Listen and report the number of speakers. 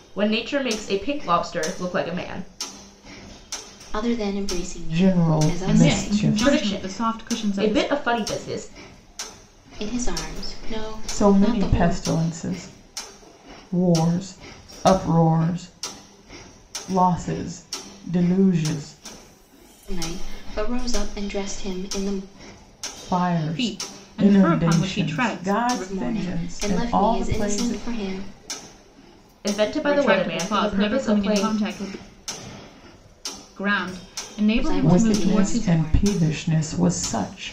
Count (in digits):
4